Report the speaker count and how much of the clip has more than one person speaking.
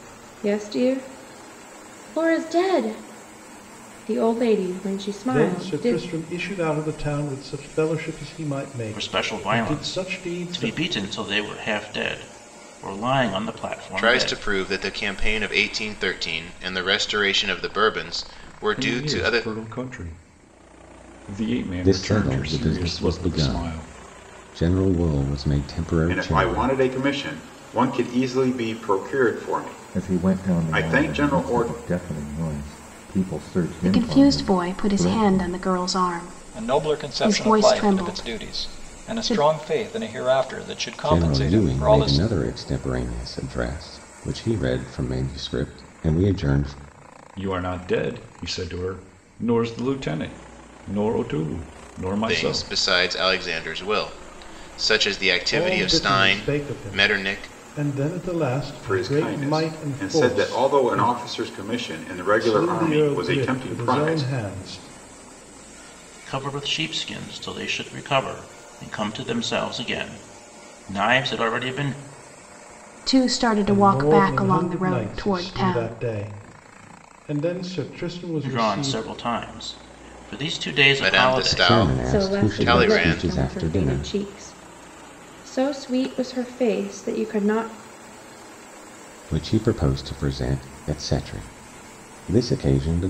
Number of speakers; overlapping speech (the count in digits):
10, about 30%